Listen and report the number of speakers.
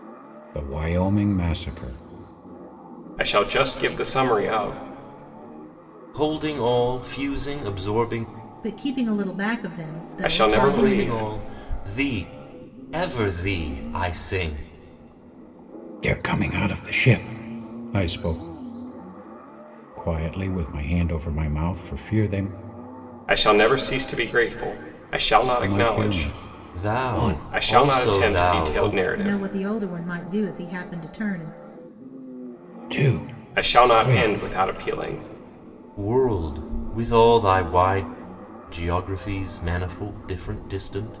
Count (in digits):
4